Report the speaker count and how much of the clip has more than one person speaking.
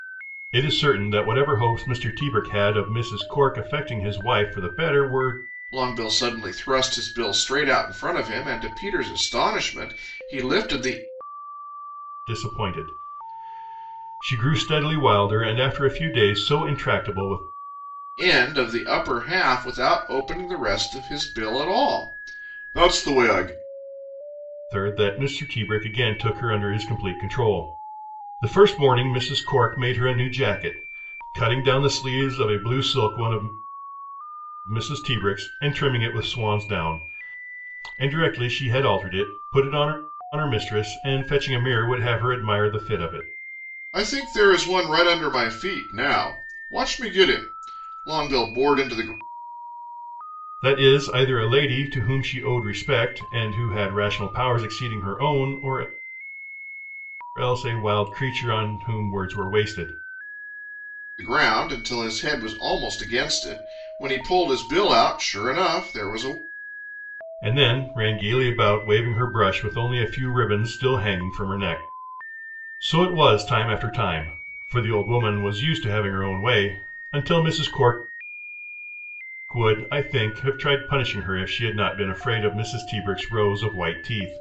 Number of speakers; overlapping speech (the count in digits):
2, no overlap